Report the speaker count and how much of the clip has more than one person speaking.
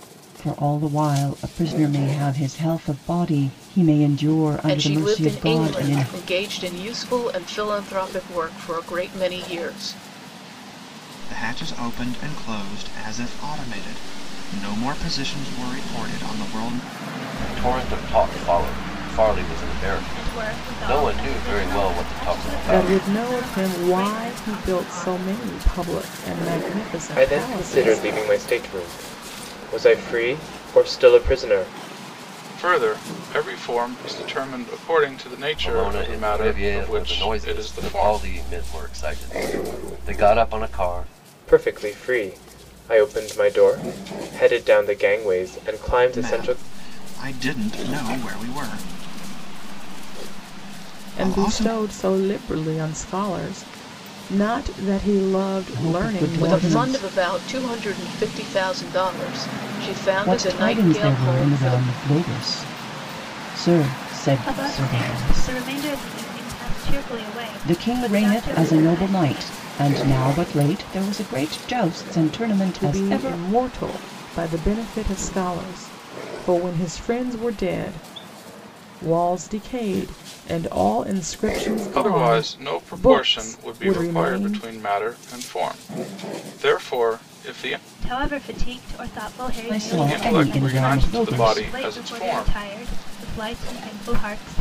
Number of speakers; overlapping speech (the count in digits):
8, about 26%